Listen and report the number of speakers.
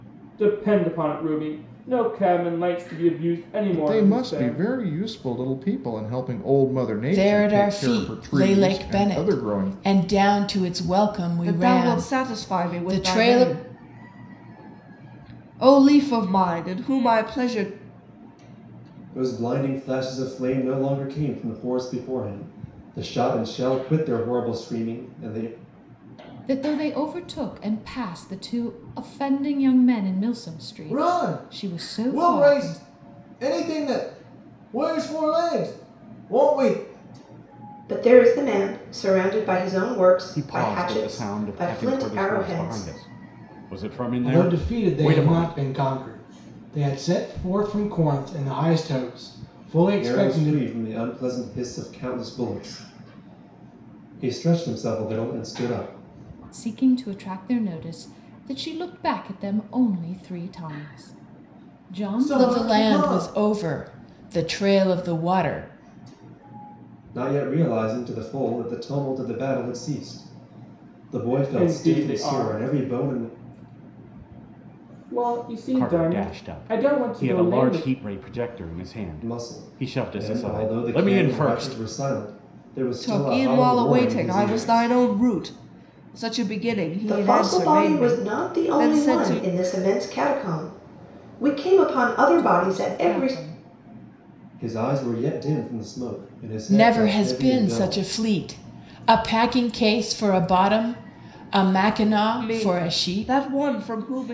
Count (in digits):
10